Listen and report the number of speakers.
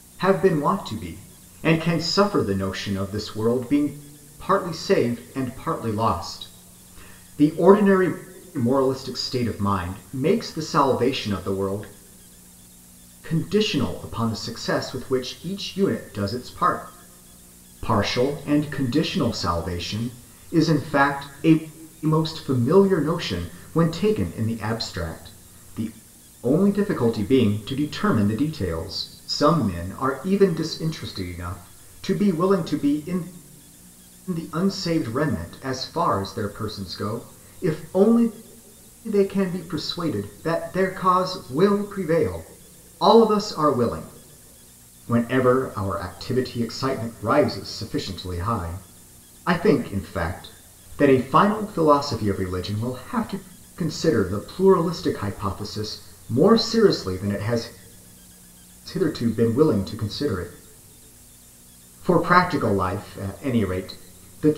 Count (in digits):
1